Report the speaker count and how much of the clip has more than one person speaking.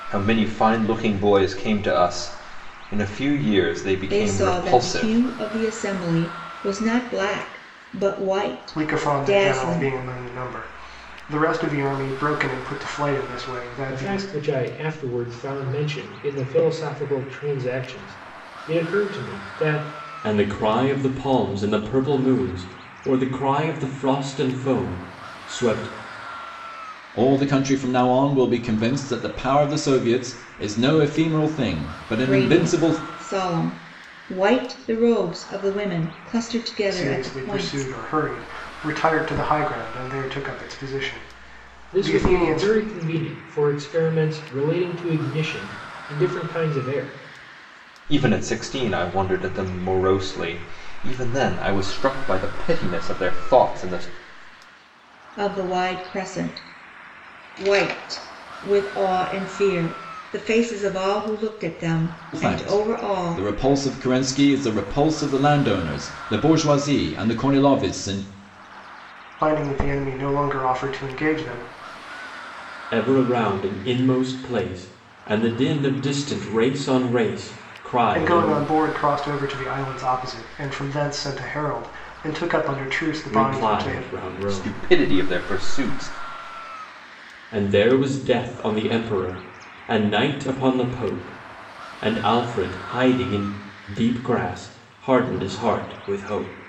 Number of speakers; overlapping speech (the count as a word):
six, about 9%